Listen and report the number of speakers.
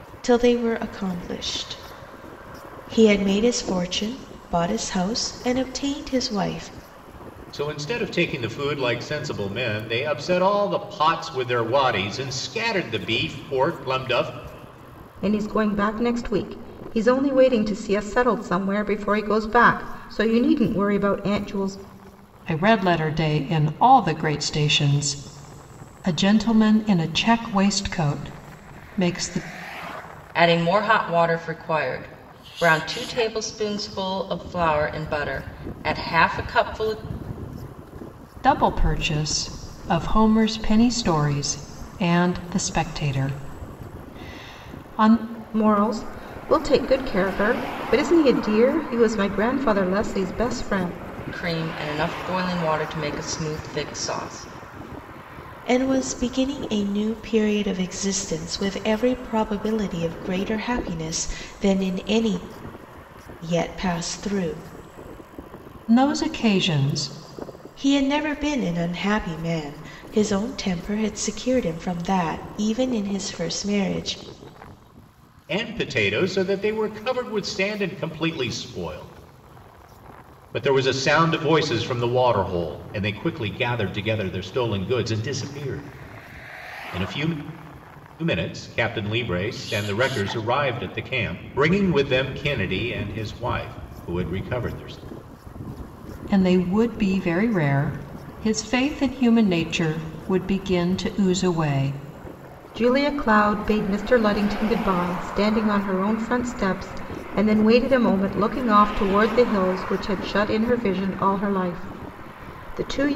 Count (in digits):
5